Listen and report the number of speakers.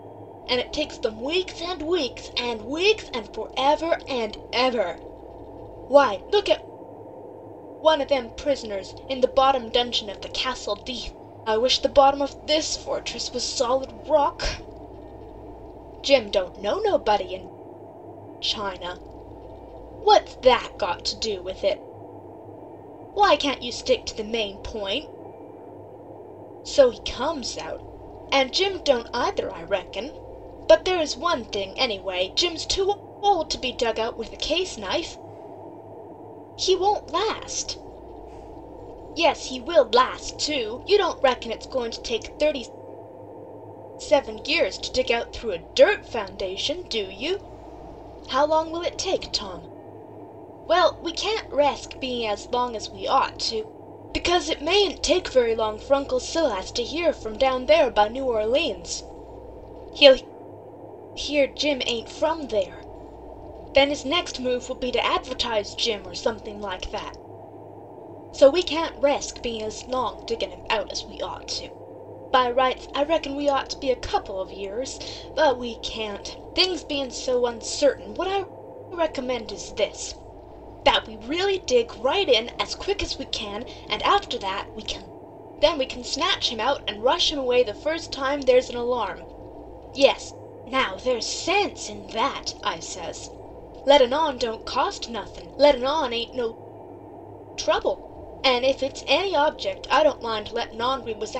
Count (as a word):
one